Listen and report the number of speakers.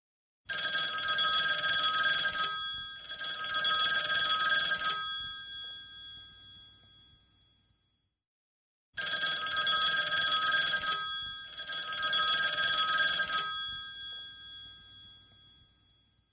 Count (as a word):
zero